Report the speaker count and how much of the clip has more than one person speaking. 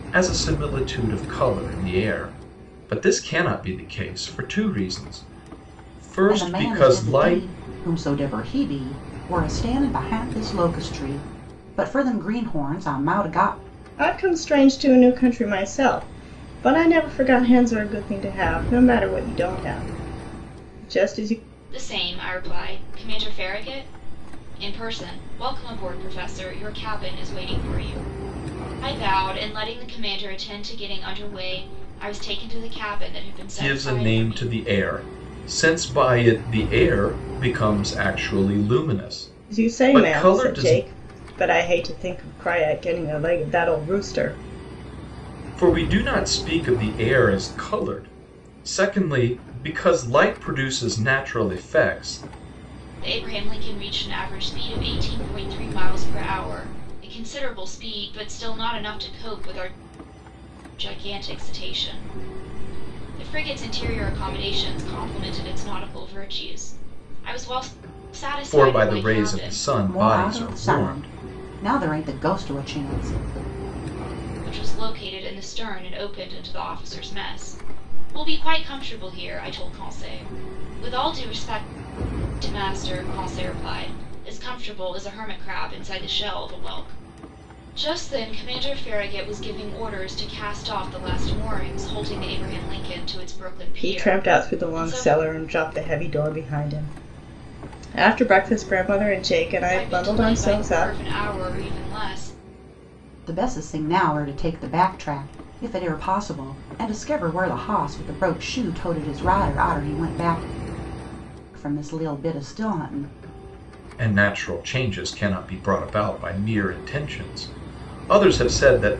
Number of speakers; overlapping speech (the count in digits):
4, about 7%